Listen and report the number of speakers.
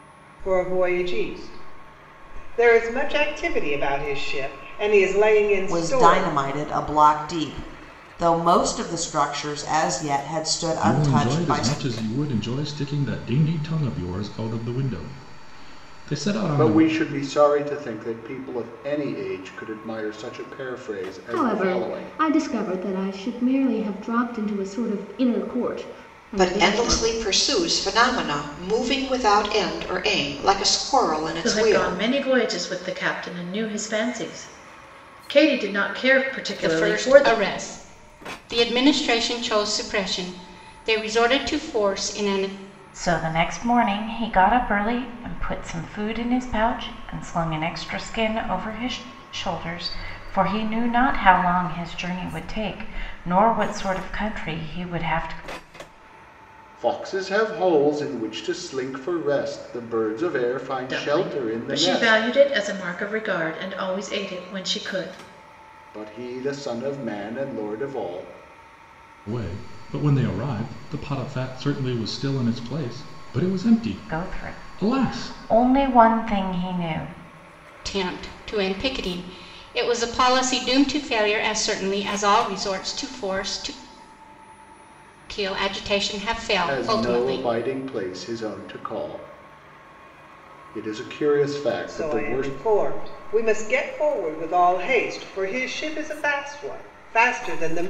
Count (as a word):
nine